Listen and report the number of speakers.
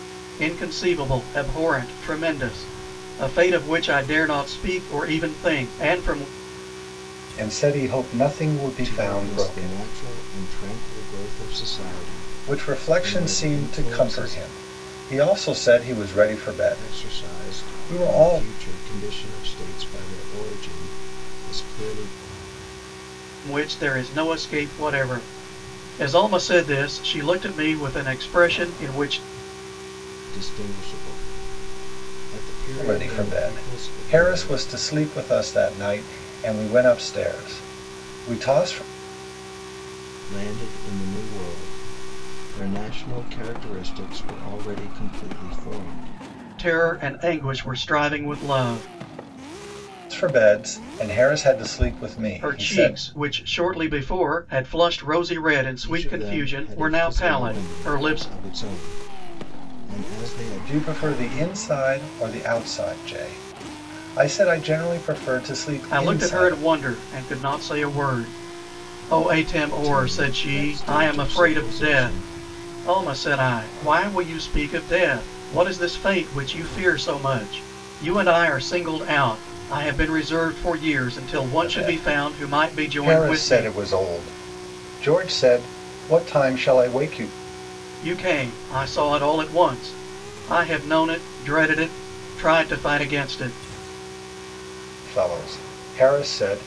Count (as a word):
three